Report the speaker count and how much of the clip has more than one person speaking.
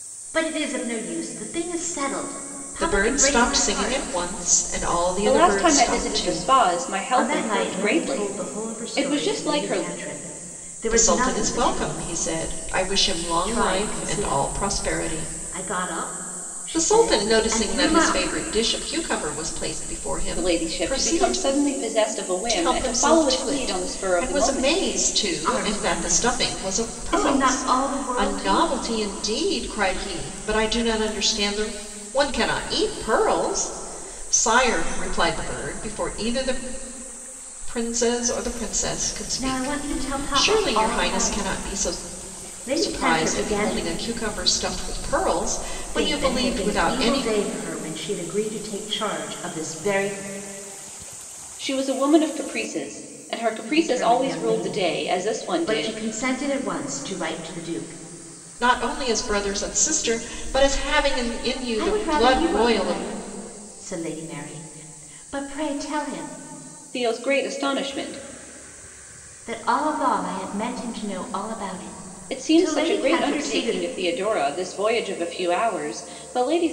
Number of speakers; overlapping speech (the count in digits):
3, about 36%